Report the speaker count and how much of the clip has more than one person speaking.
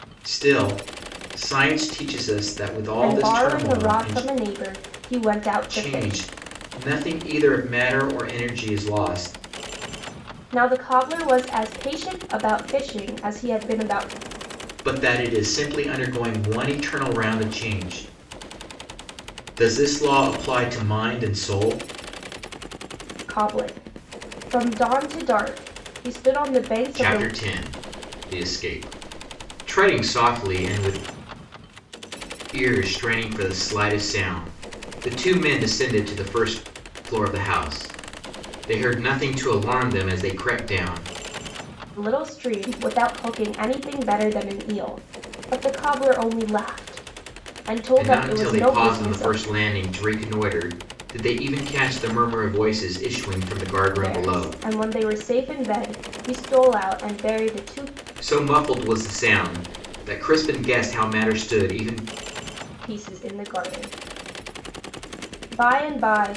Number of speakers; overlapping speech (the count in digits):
2, about 7%